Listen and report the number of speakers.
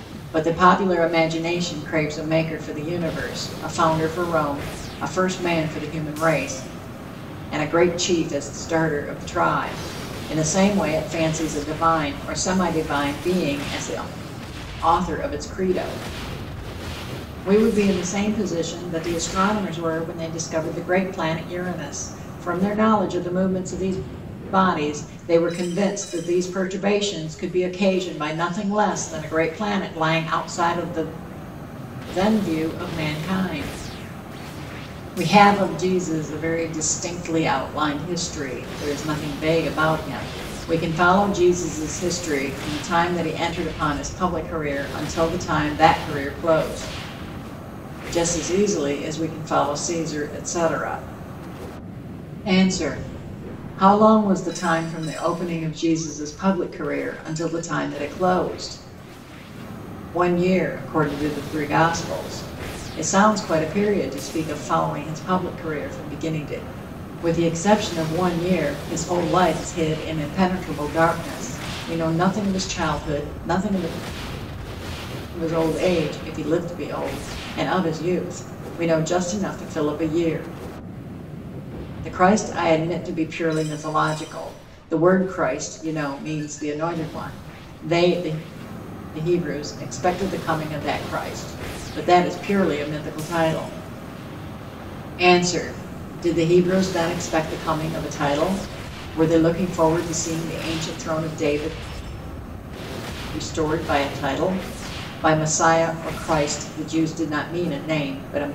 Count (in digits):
1